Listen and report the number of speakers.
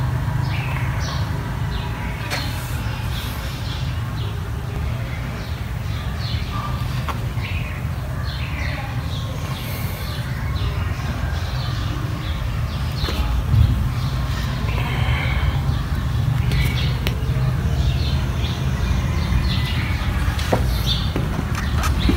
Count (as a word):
zero